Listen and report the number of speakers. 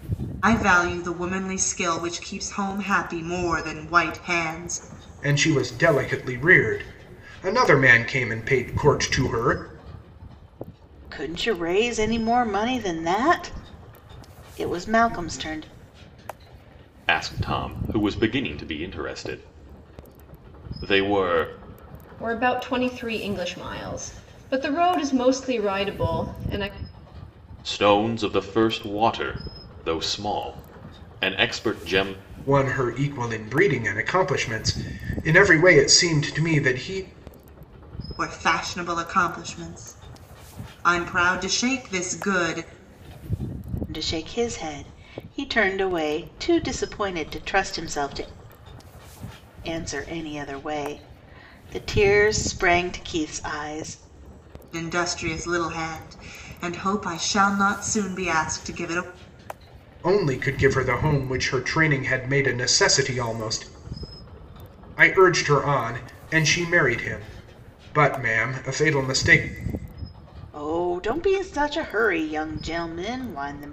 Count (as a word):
five